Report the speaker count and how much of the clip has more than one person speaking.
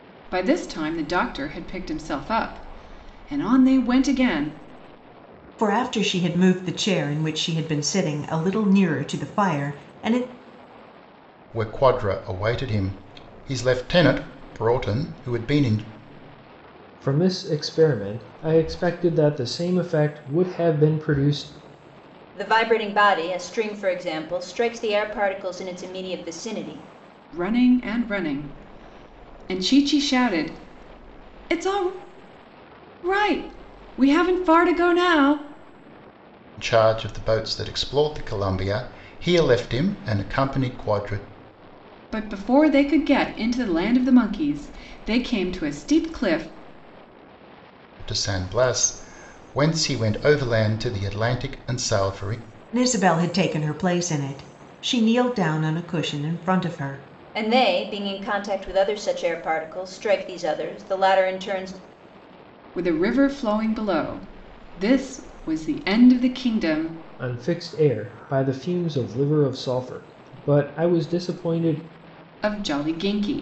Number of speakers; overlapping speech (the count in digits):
5, no overlap